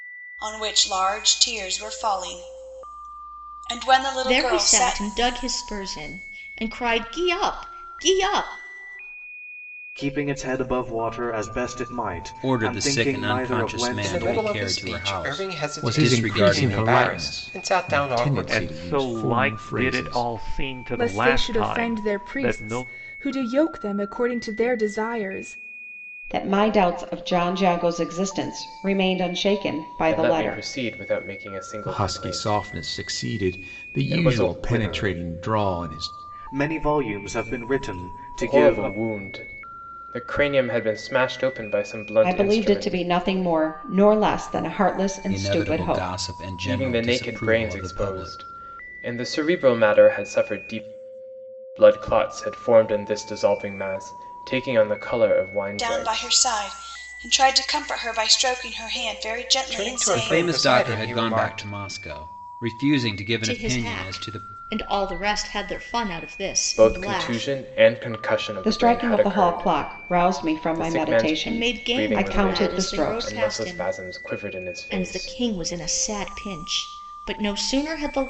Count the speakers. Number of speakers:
ten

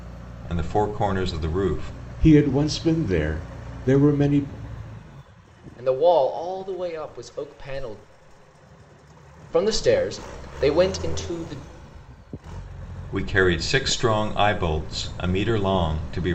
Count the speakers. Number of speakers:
three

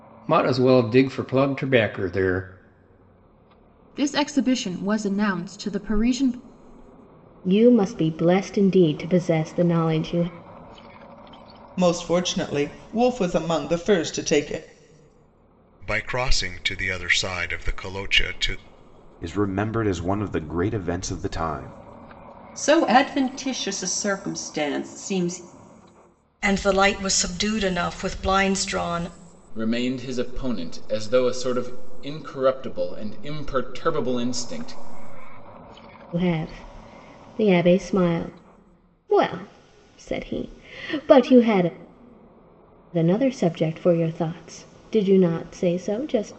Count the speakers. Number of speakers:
nine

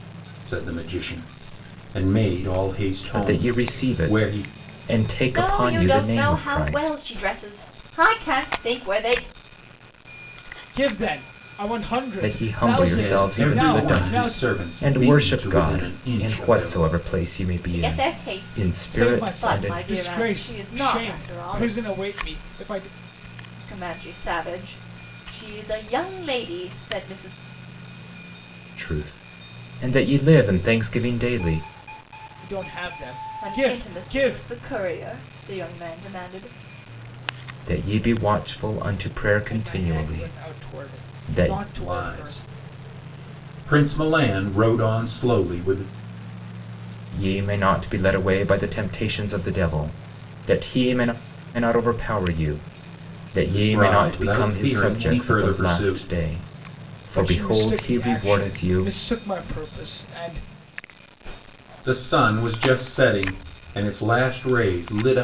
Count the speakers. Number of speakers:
four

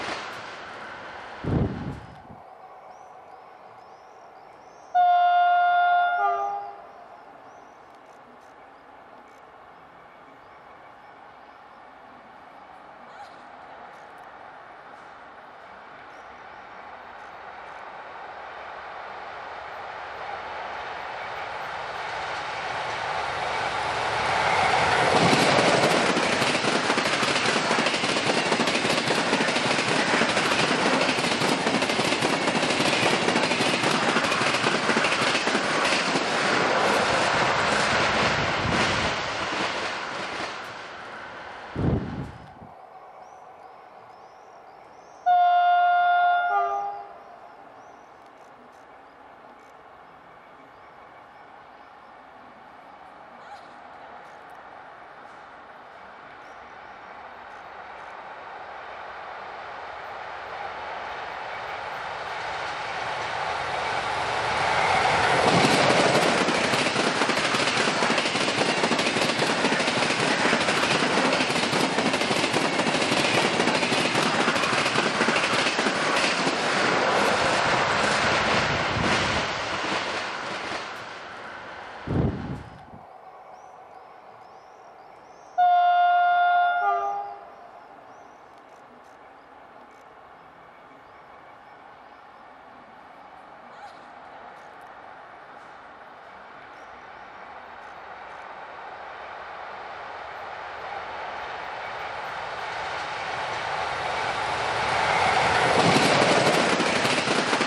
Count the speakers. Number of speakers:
zero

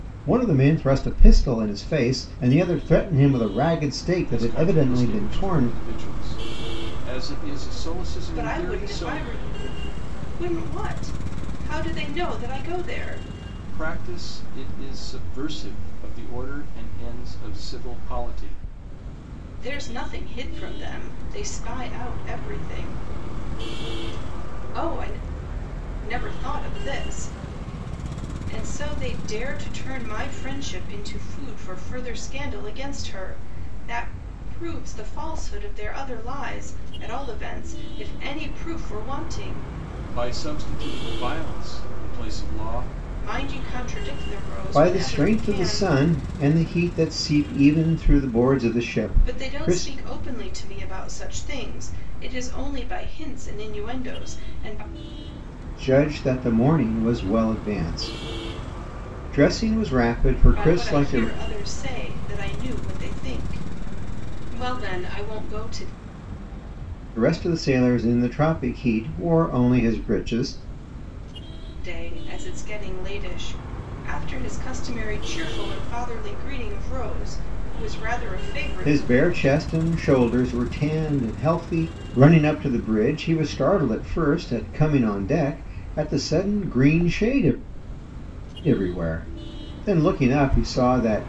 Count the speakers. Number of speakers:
three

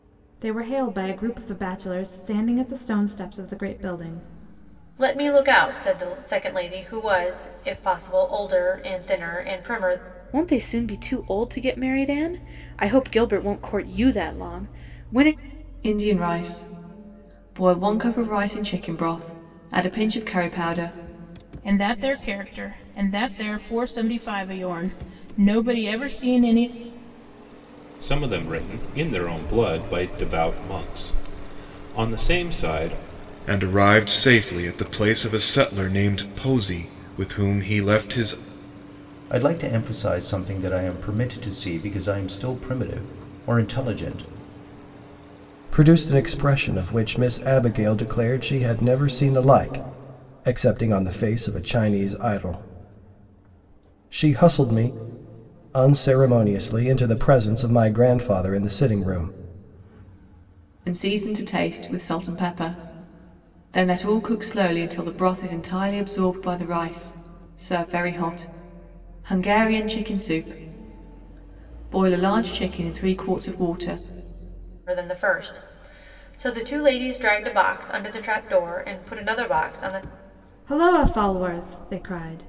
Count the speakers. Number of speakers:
nine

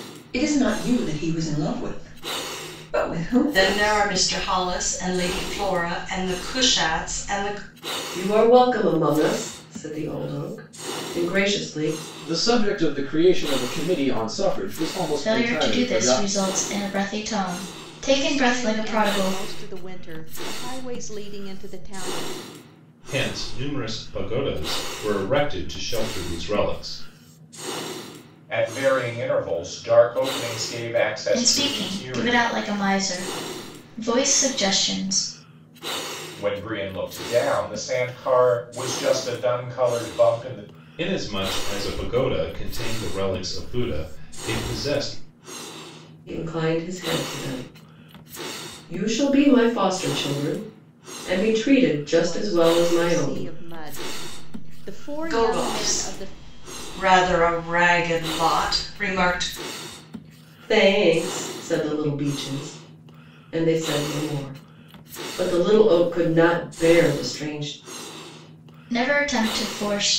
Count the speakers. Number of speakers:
eight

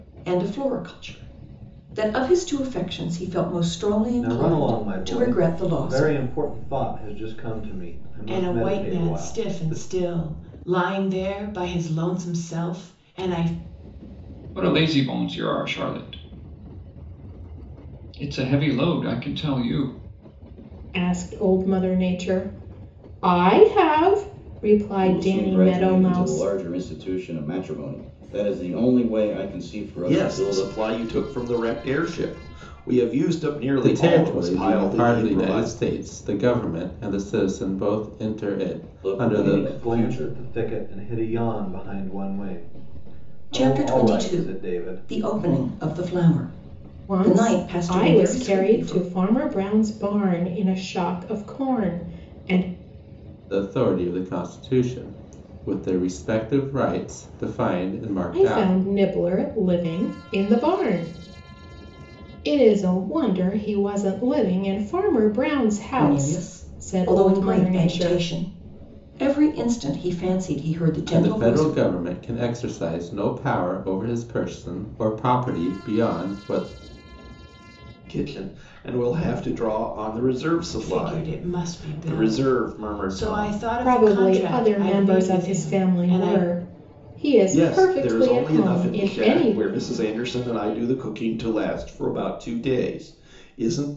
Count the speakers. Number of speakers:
eight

